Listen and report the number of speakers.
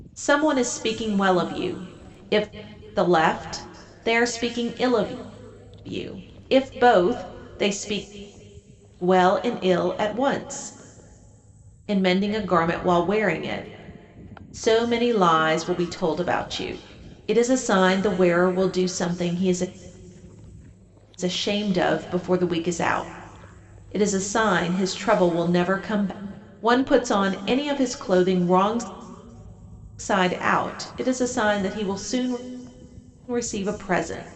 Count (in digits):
1